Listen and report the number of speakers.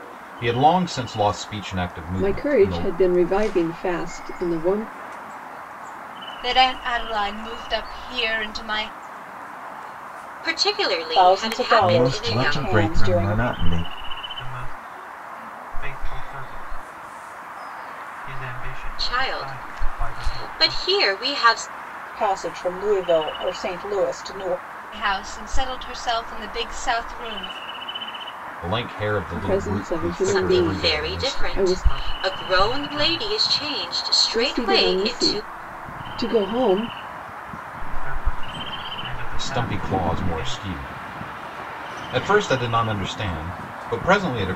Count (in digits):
7